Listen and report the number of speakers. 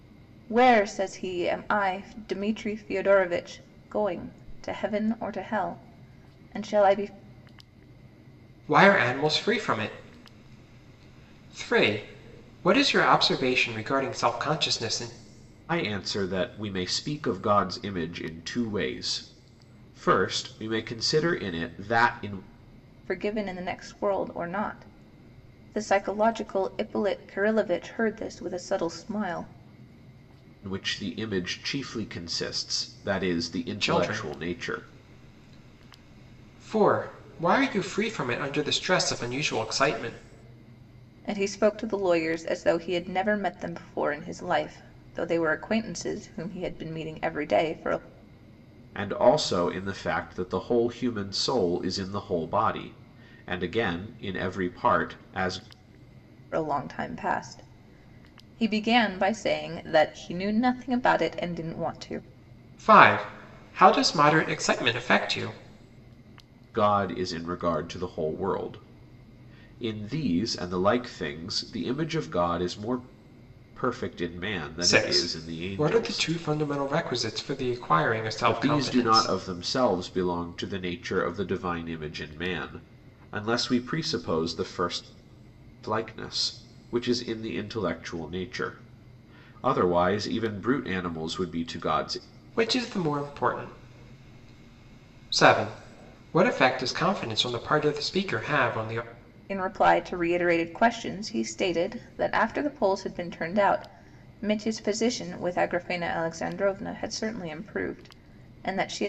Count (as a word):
three